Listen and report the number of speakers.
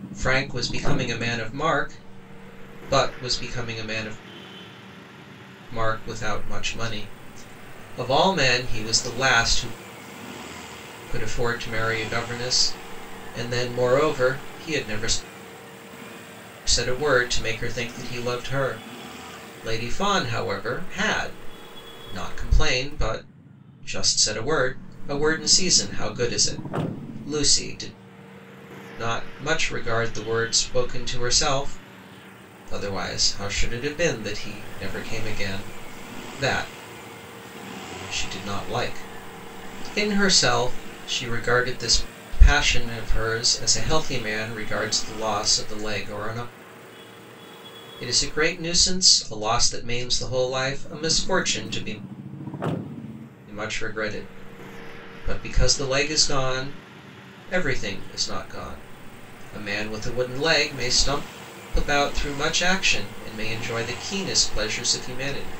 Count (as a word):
one